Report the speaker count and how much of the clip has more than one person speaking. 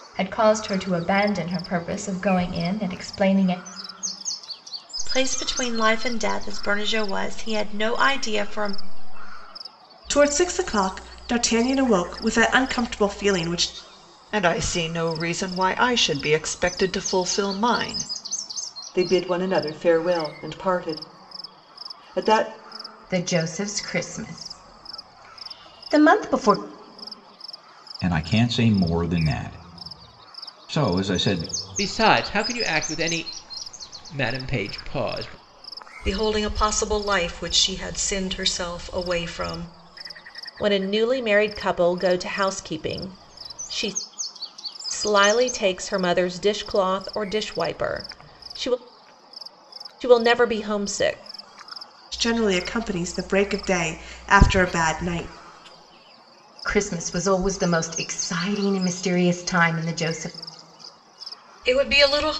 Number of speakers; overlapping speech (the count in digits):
10, no overlap